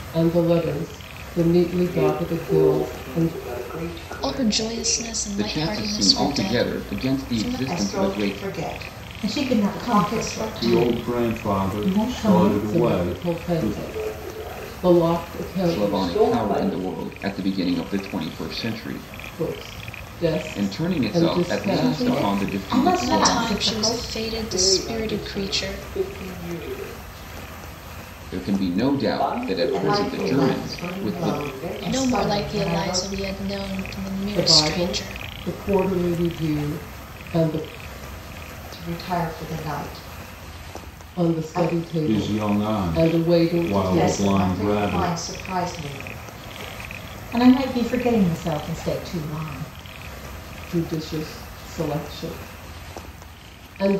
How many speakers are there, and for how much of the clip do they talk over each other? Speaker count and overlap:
7, about 50%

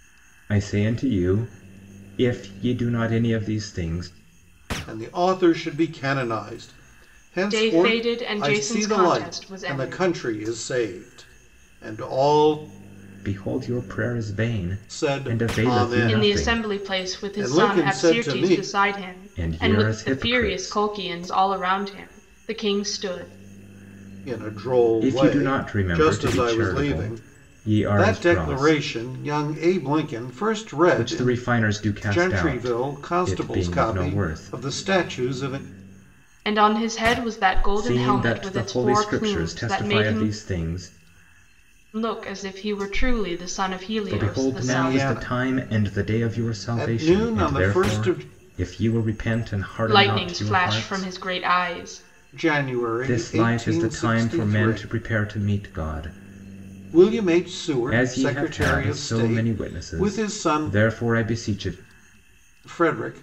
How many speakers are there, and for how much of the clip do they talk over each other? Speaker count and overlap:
3, about 42%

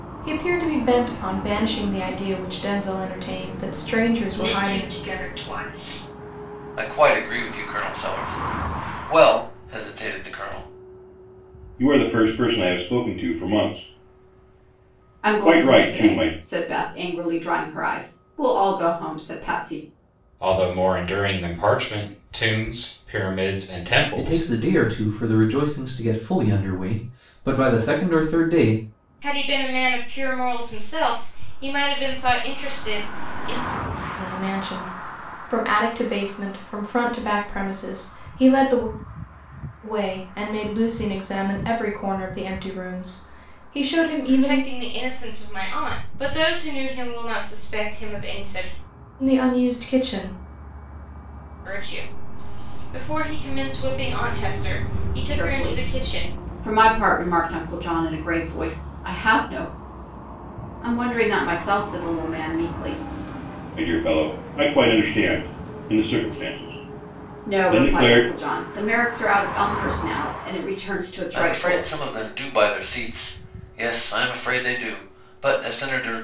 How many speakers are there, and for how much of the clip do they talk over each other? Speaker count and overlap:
8, about 7%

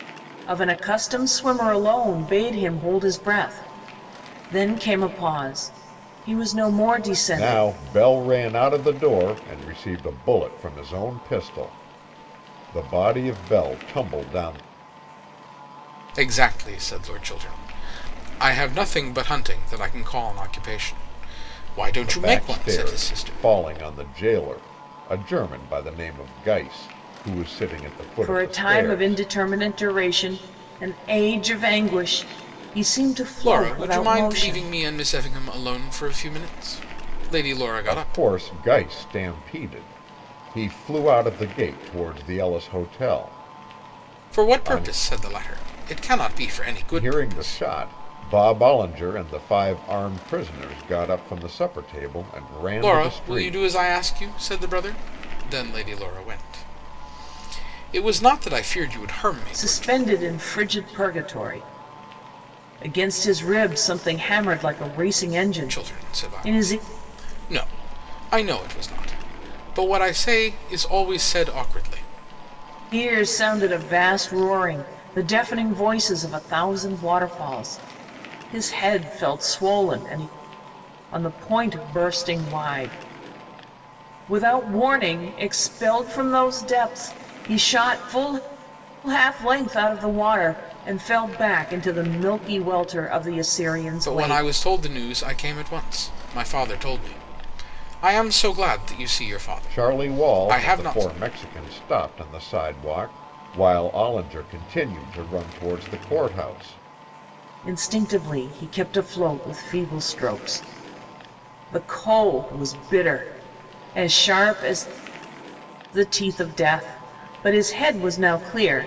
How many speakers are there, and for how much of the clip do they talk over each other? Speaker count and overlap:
3, about 9%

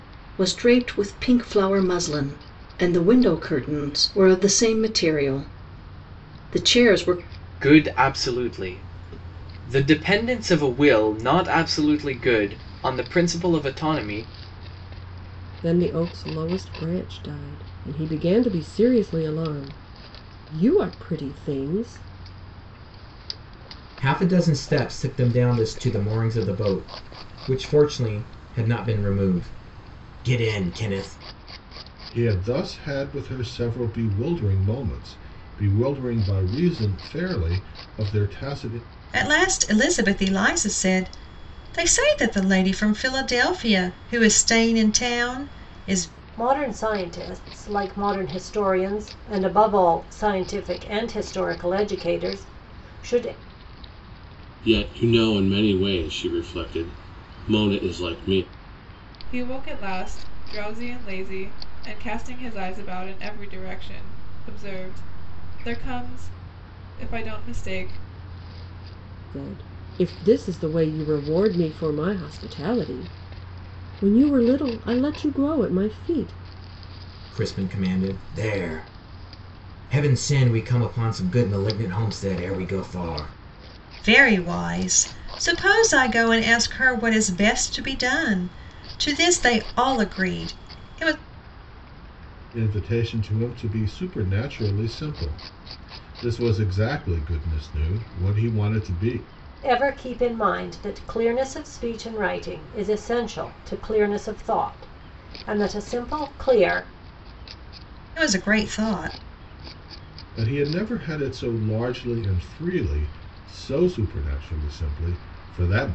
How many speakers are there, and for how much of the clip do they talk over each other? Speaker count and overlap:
9, no overlap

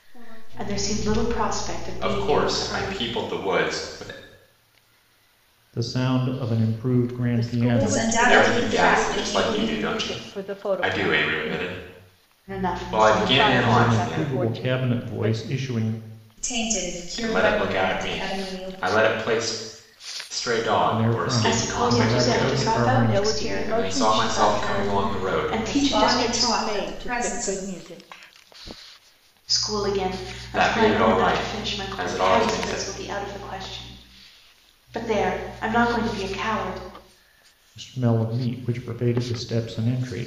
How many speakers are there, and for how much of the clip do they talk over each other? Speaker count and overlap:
6, about 48%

